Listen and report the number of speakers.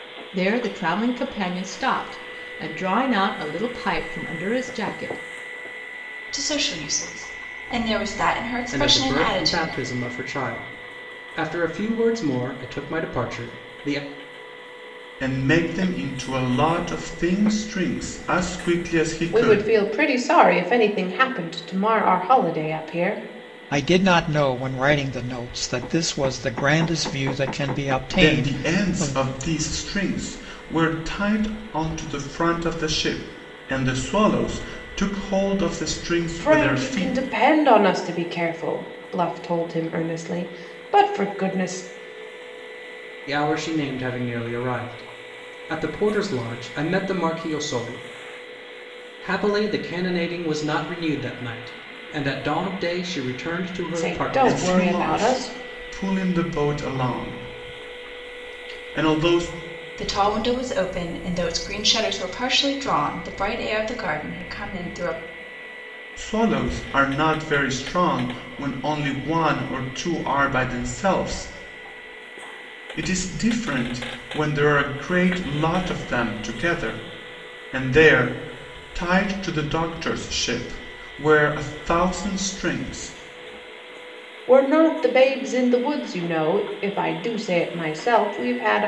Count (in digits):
6